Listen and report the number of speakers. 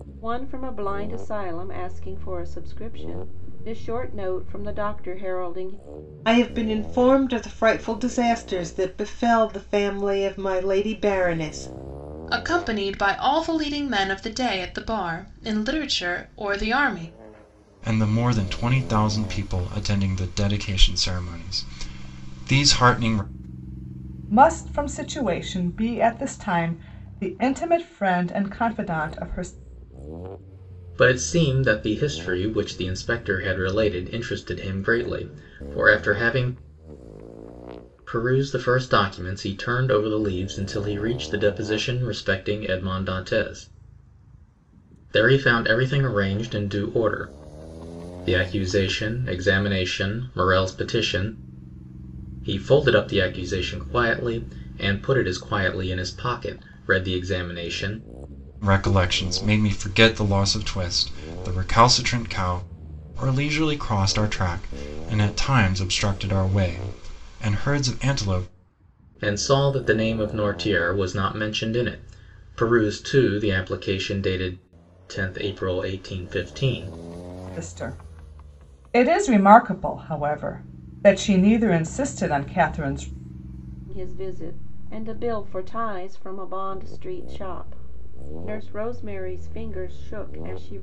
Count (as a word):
six